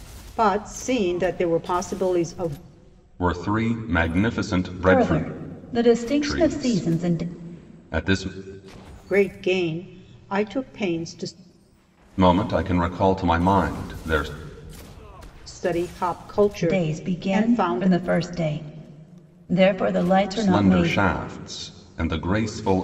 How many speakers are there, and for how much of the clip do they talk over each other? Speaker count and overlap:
three, about 16%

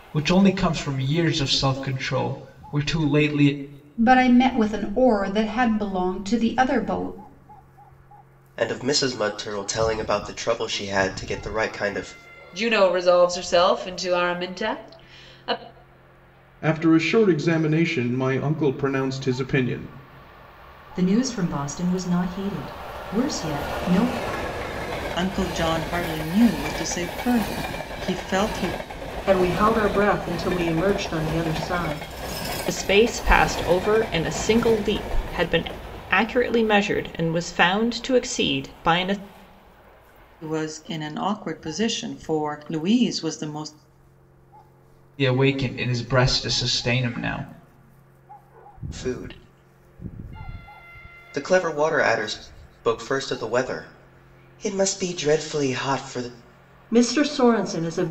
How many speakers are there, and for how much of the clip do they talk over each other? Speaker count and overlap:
nine, no overlap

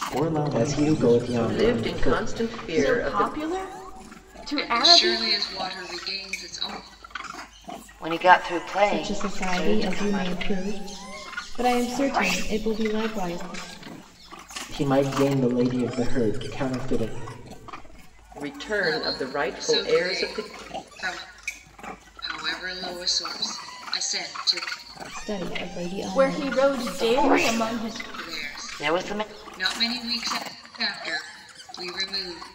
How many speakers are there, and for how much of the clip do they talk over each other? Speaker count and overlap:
seven, about 30%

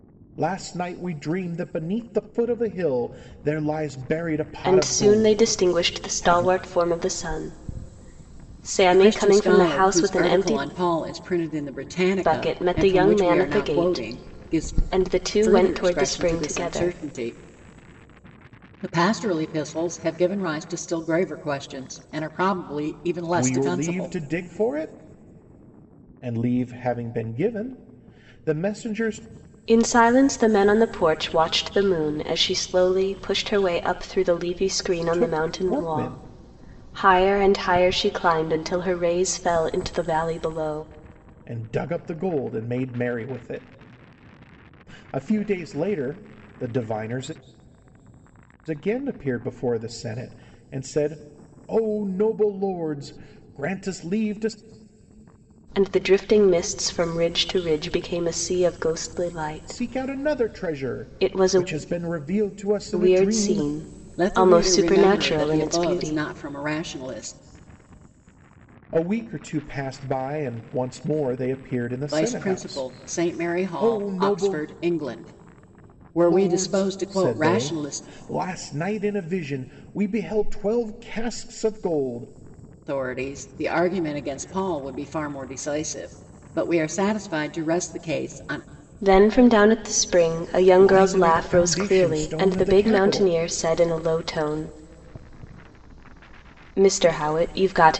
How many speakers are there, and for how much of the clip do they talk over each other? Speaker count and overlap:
three, about 22%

